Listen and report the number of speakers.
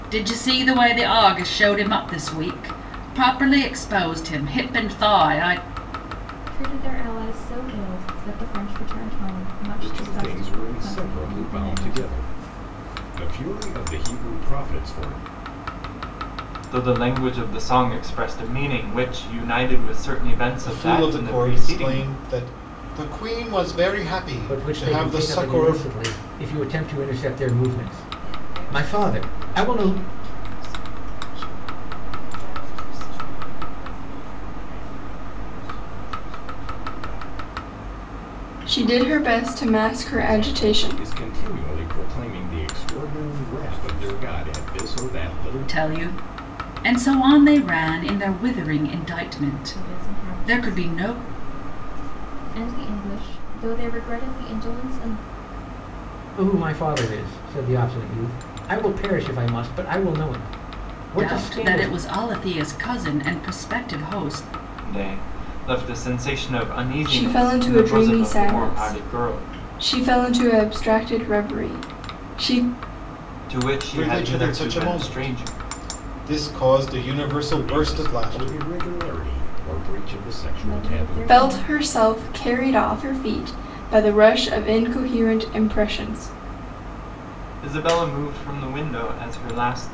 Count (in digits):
9